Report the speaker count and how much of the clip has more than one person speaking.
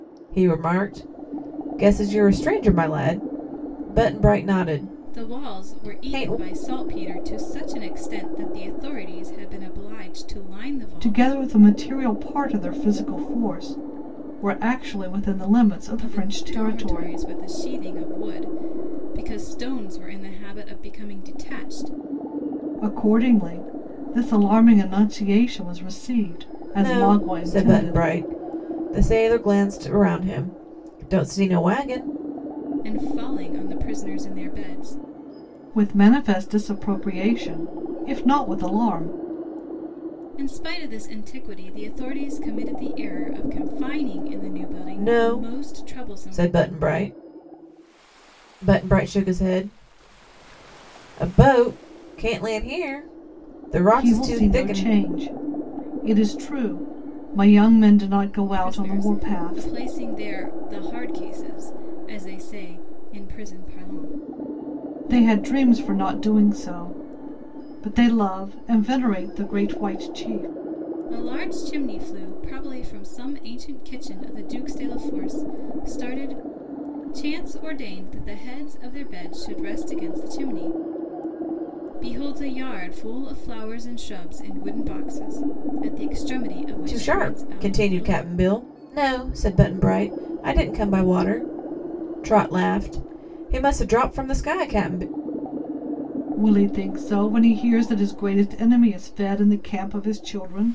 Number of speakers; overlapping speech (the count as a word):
three, about 9%